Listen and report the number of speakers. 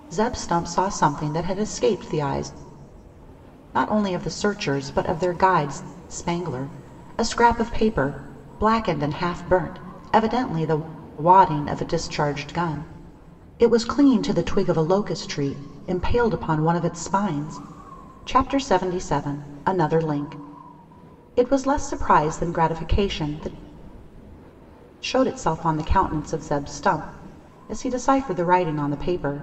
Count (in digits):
1